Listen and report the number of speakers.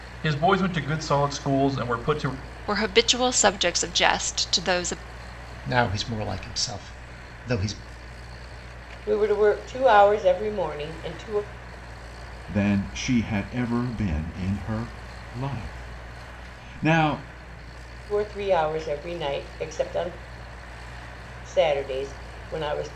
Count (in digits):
5